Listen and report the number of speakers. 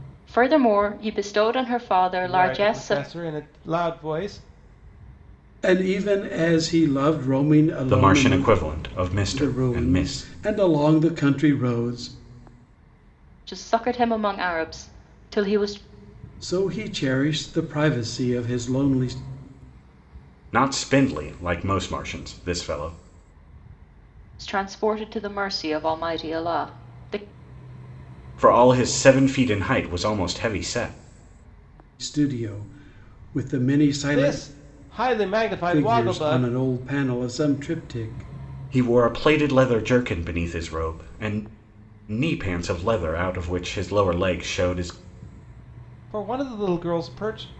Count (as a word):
four